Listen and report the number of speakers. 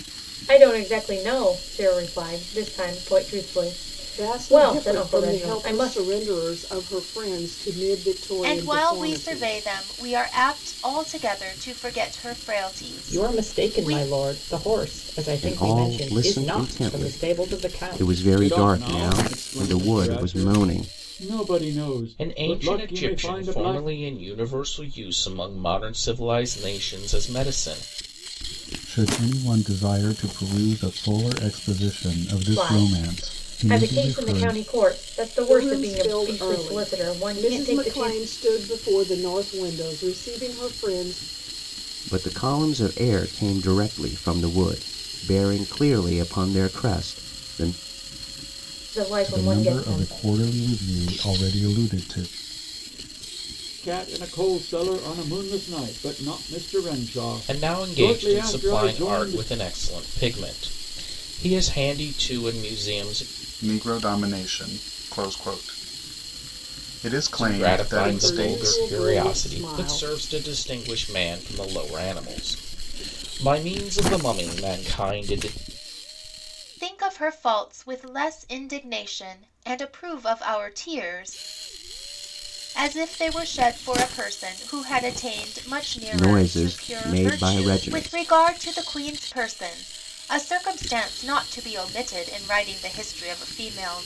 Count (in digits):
8